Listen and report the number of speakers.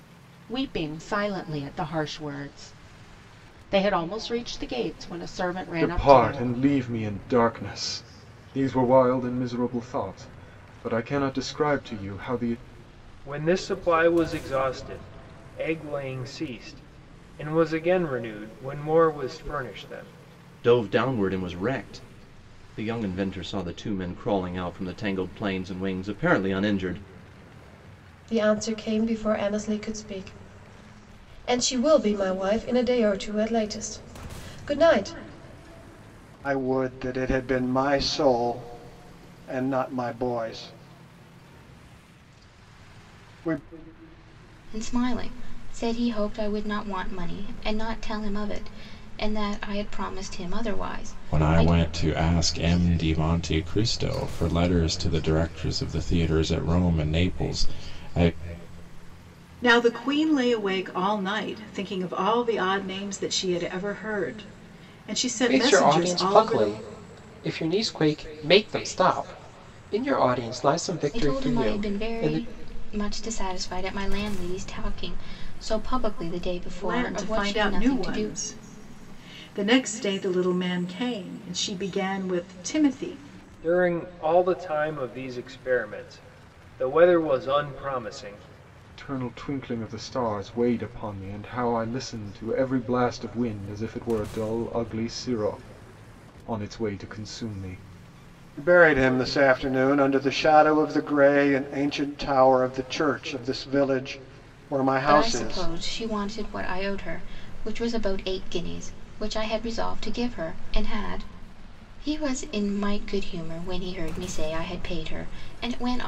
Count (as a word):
ten